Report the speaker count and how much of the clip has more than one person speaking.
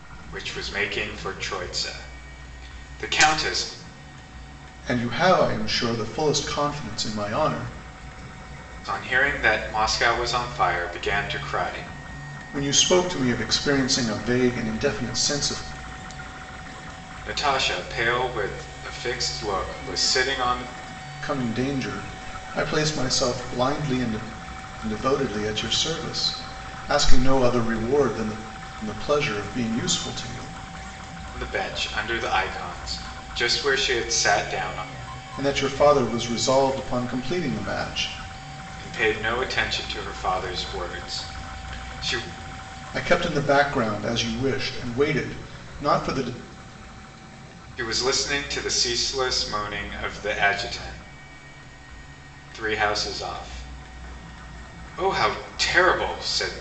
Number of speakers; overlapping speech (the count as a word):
two, no overlap